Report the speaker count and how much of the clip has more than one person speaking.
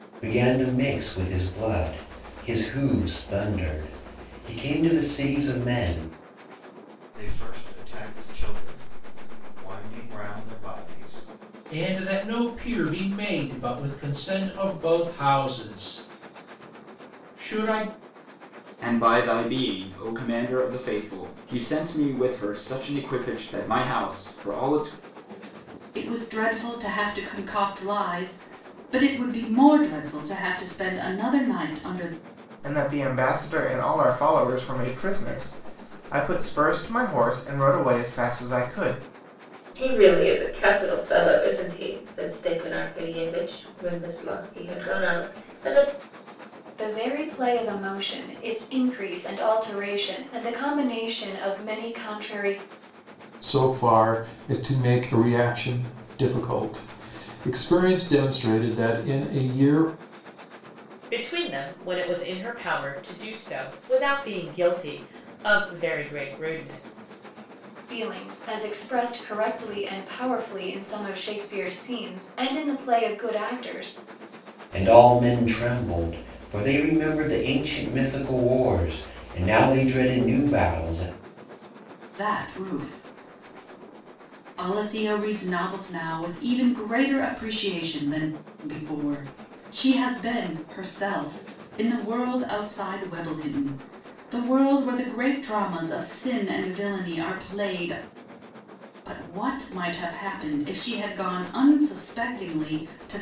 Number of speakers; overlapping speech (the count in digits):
10, no overlap